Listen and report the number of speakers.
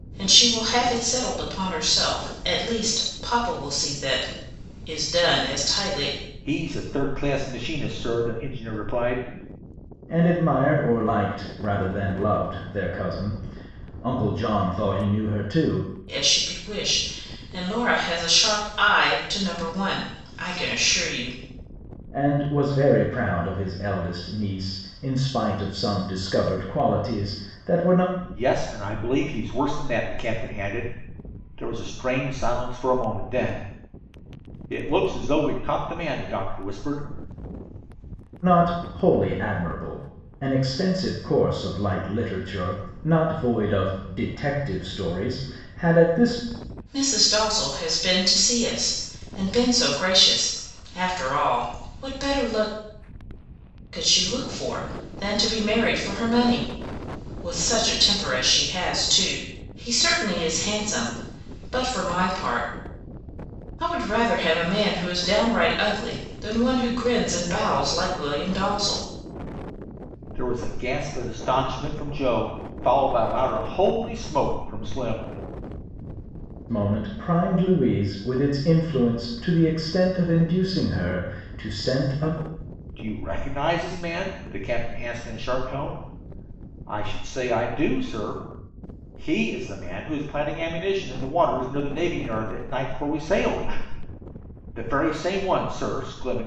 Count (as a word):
three